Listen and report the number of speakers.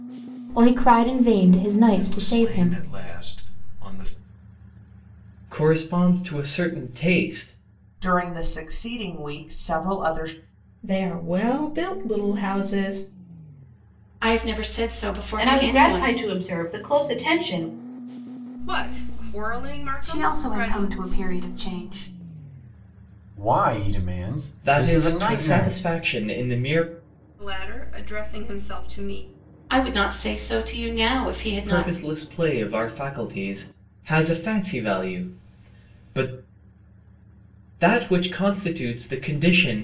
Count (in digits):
10